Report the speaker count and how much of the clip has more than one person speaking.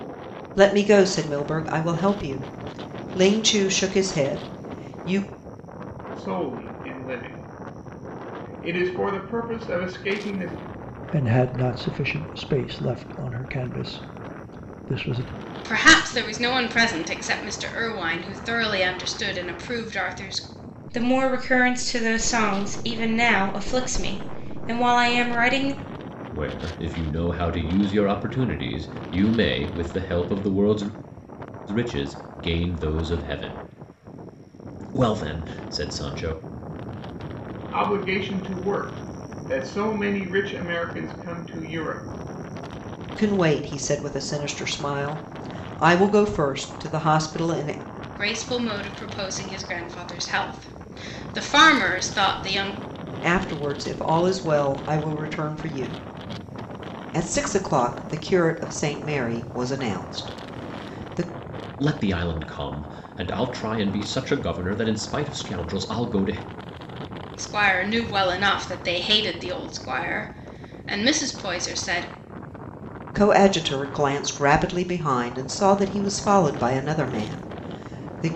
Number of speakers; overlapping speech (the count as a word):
six, no overlap